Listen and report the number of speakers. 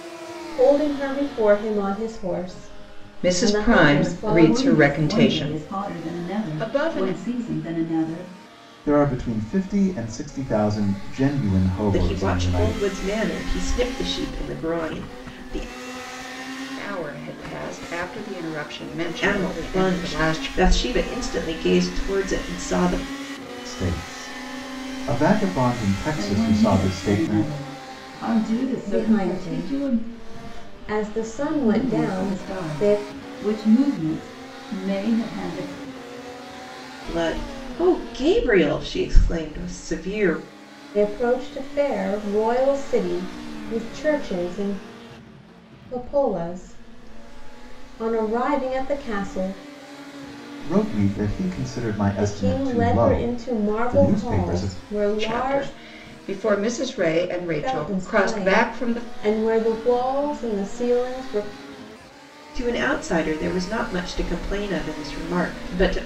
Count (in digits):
5